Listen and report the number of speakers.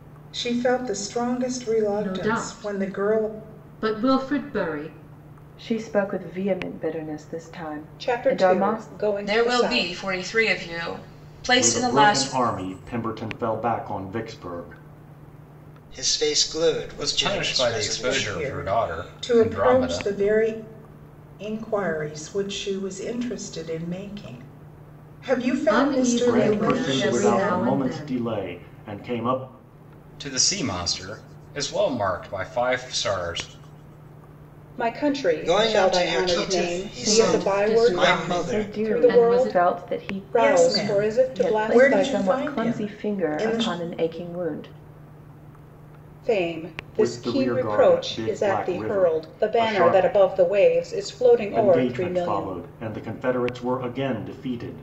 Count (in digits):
8